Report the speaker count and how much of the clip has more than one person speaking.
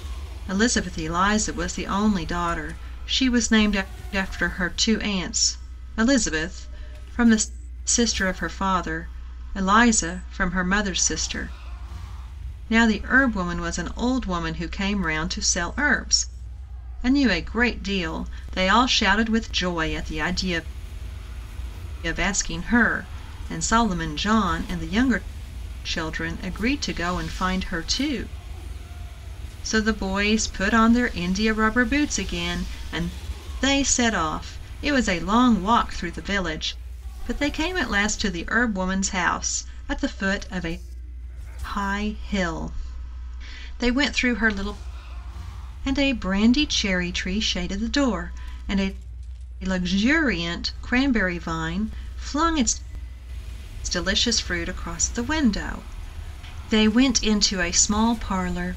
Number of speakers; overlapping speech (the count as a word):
one, no overlap